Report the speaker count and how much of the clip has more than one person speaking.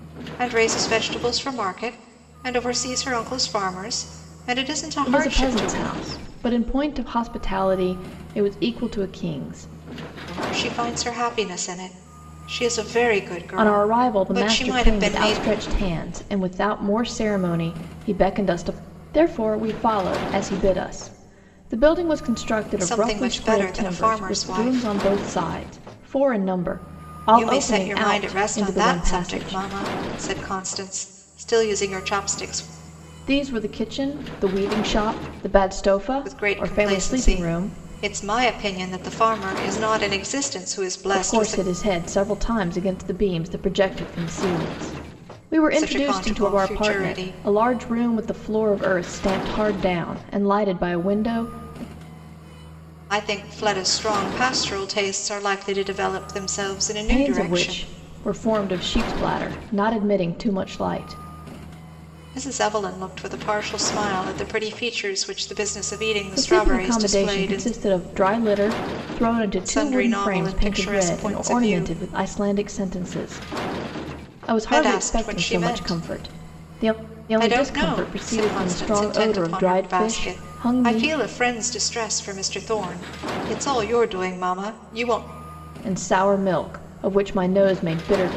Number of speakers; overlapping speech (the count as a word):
two, about 25%